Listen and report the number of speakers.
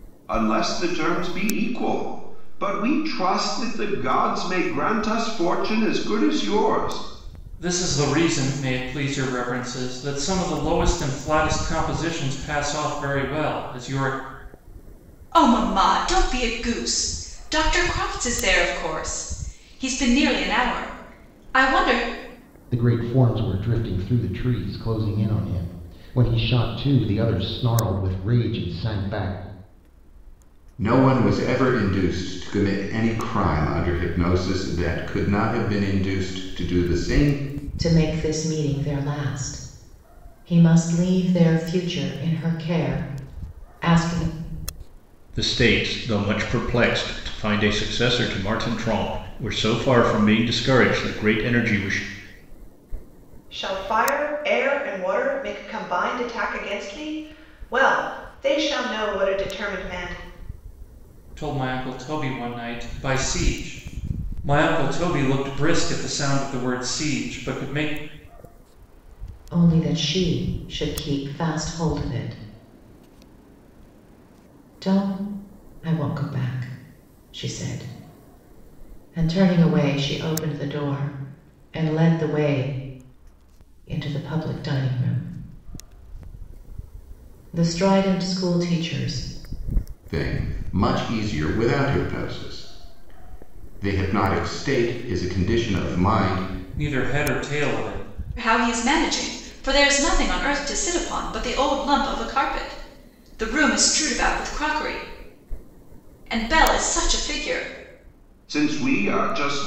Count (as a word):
eight